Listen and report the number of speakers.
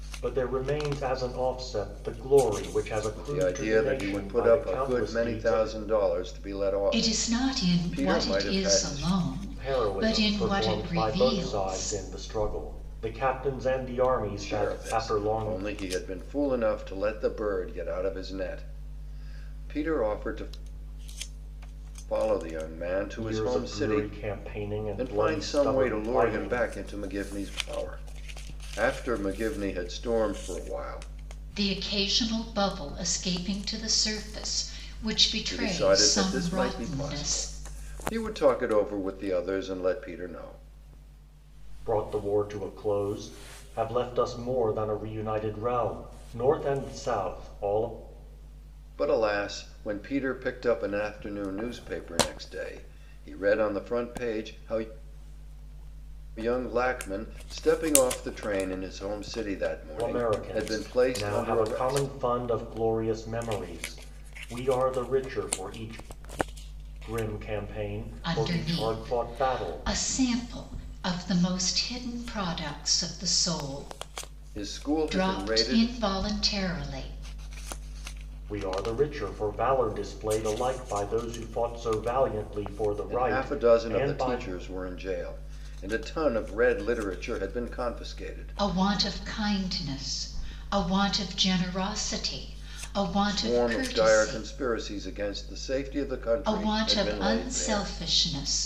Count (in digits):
3